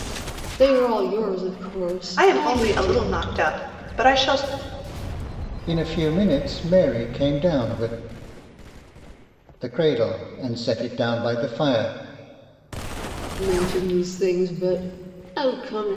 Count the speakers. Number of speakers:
3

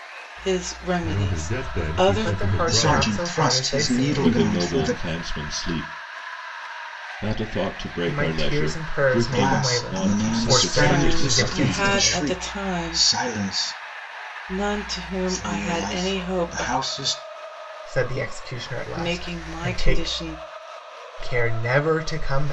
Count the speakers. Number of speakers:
5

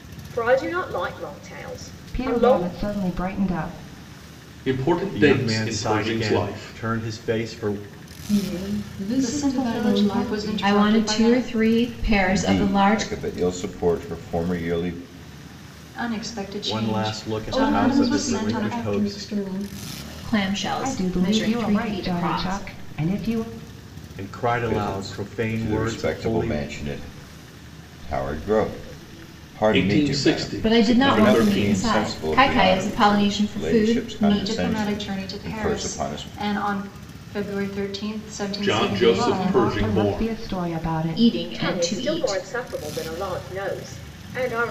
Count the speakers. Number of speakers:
8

